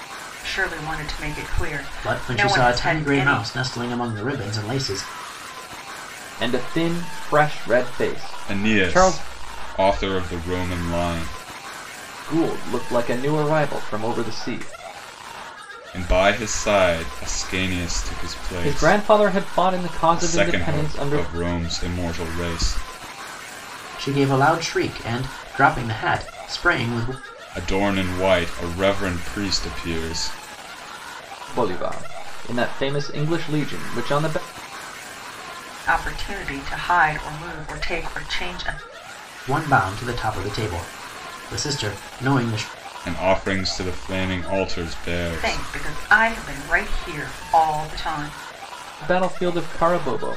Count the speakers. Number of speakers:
4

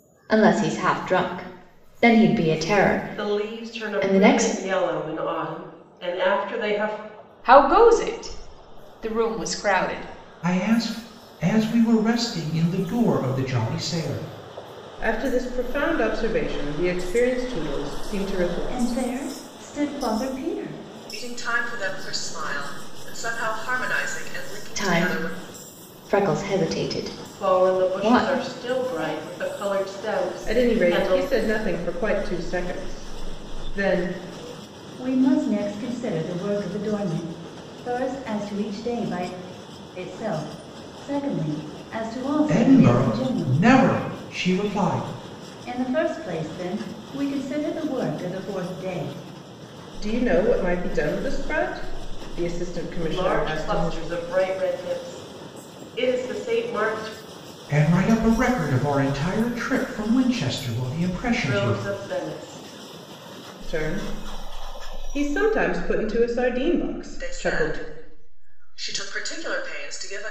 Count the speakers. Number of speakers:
7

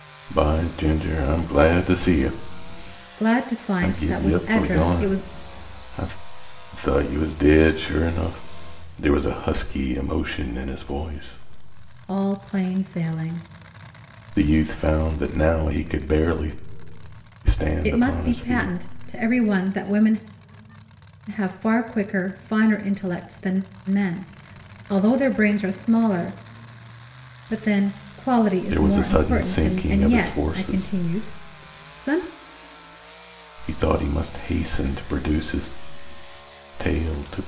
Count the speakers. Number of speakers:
2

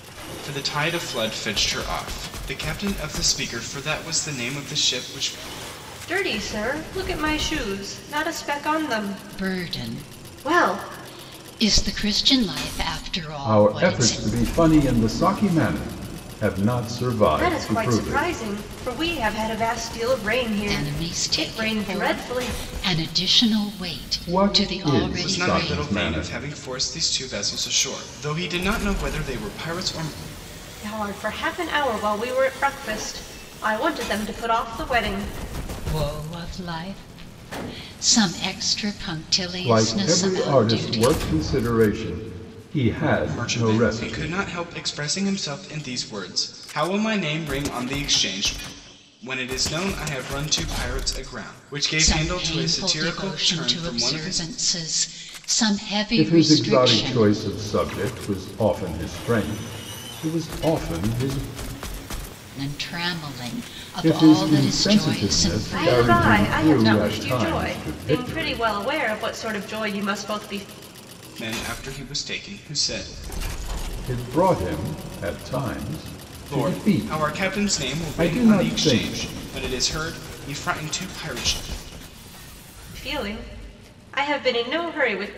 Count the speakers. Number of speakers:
4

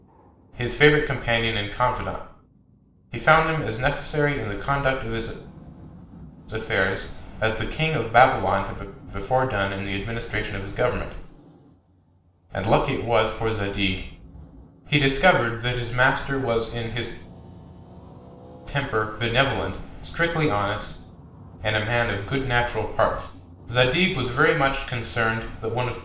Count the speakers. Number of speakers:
1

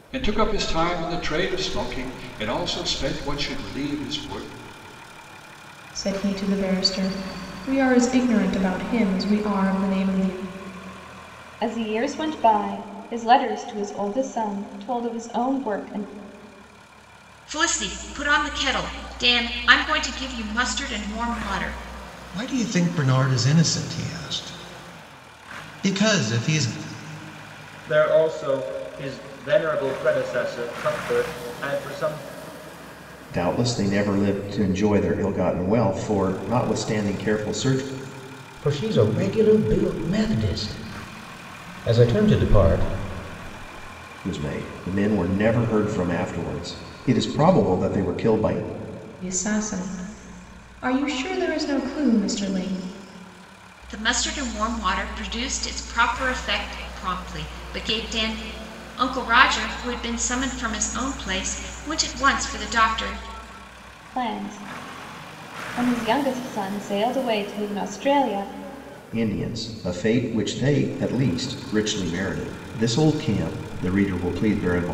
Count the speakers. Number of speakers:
8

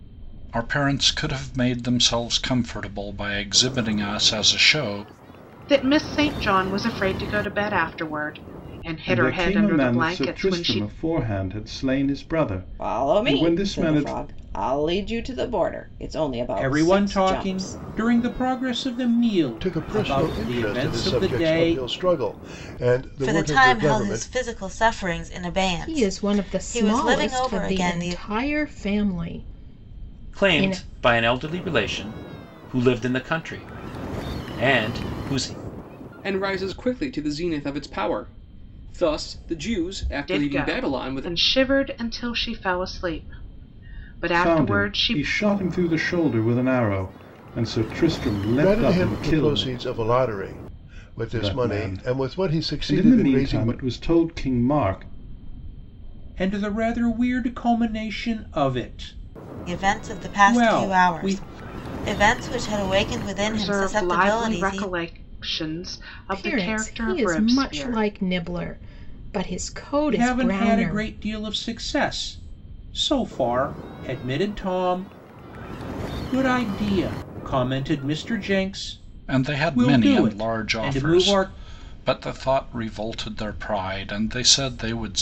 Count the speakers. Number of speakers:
10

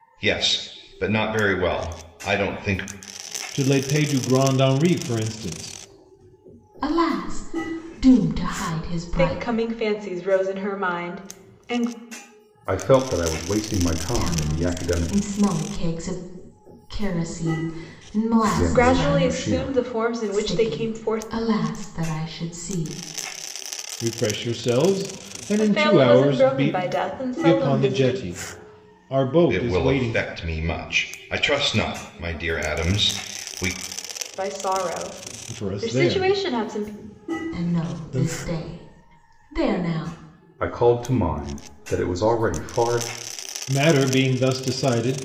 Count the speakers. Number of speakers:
5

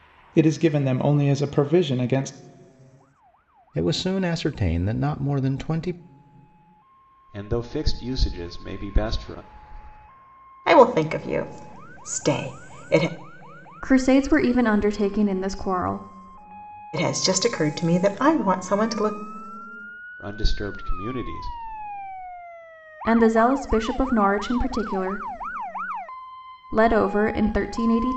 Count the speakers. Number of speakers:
5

